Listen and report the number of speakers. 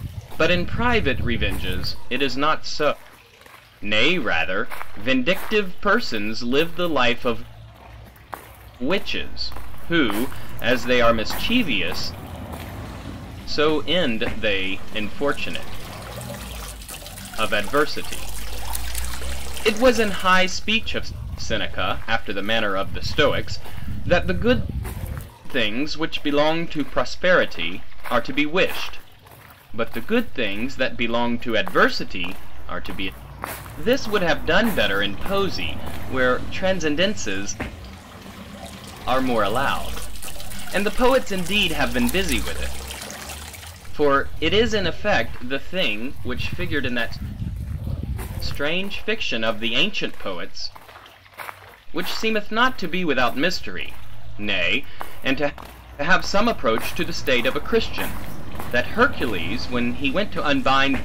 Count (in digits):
1